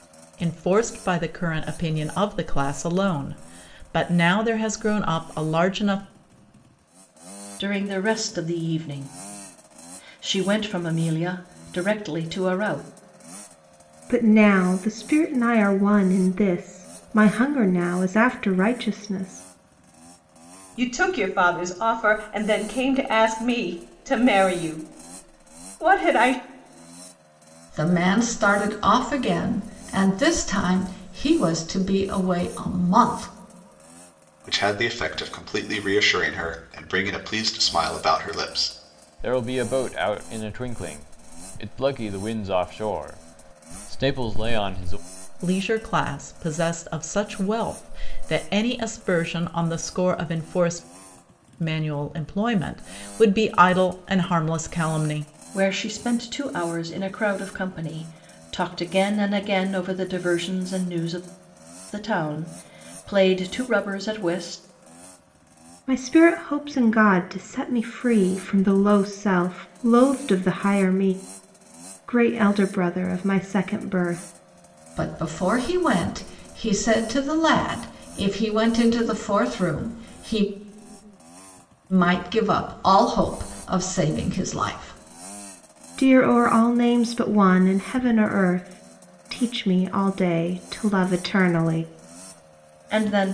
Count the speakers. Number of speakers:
7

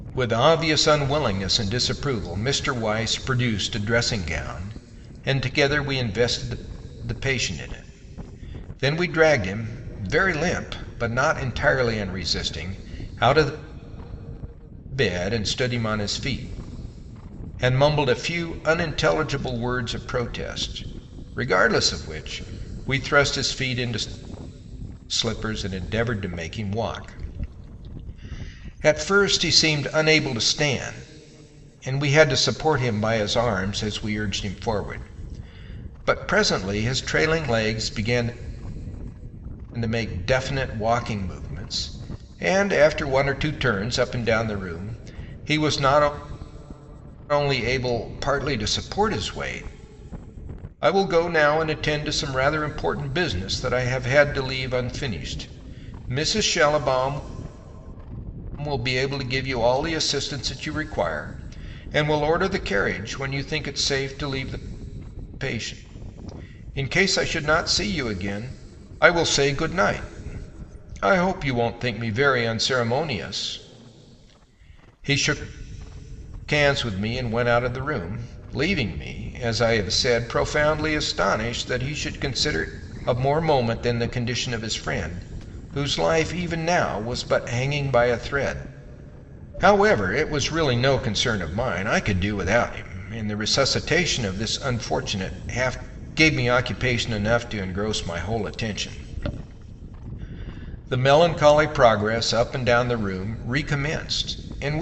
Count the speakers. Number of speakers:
1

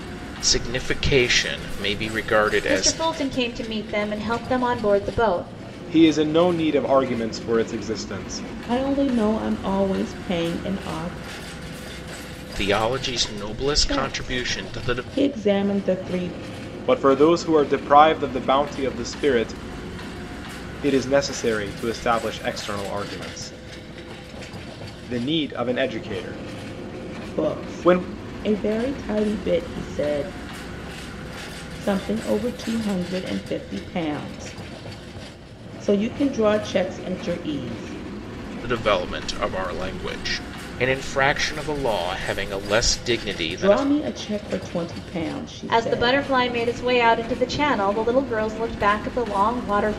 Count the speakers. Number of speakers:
4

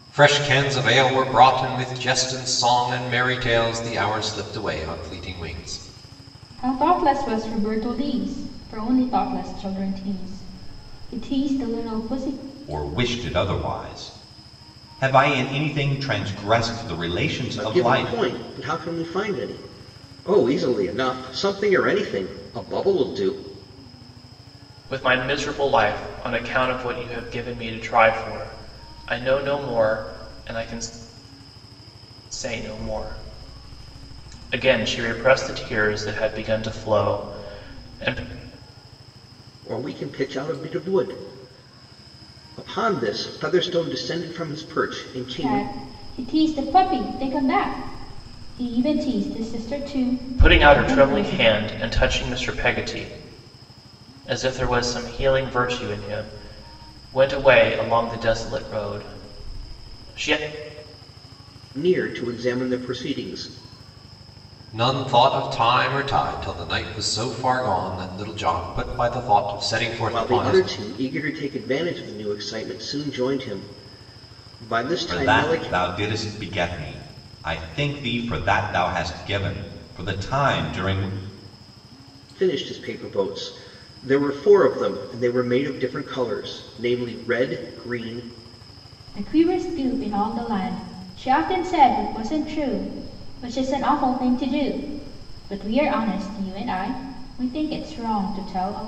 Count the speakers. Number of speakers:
5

